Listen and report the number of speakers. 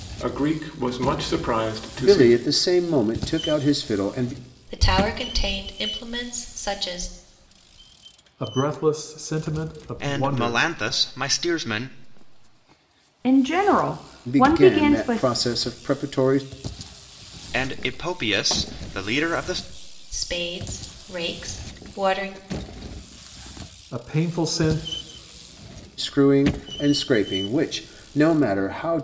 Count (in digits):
6